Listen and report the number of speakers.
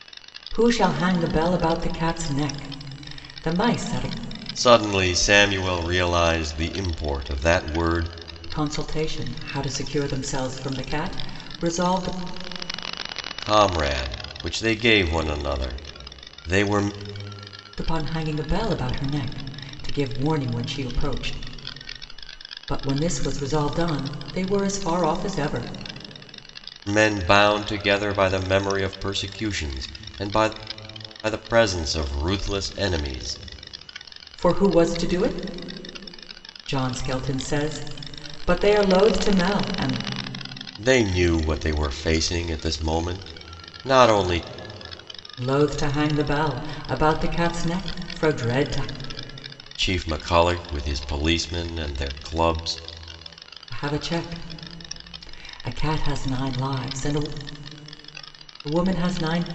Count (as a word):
two